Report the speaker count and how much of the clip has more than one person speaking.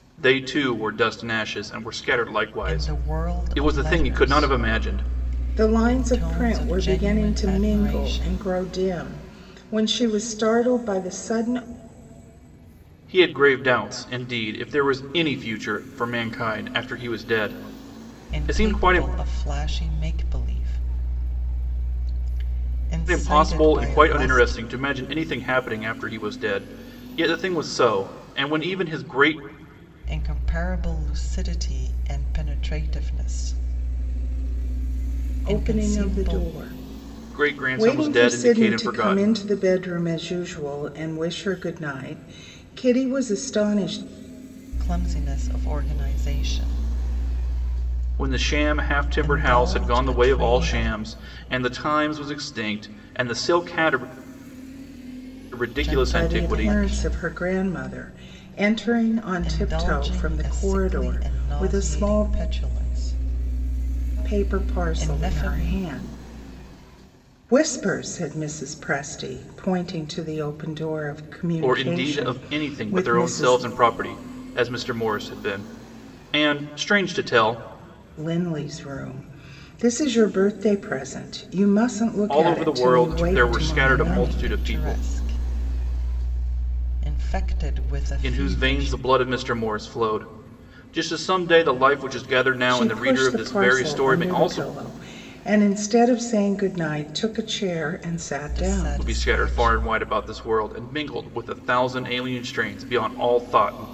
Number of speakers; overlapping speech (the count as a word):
three, about 27%